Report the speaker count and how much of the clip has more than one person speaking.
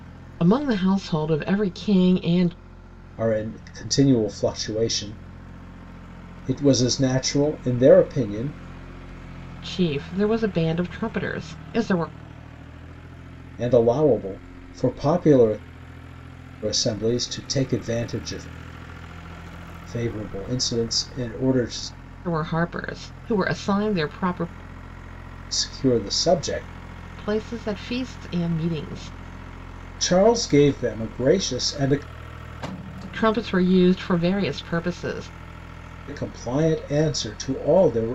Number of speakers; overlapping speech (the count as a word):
two, no overlap